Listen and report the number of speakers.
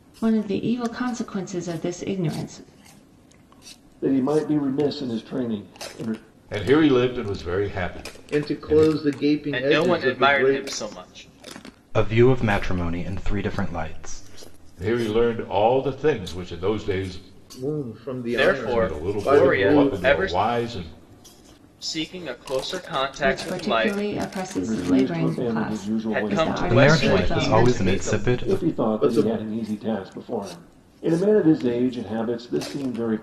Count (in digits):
6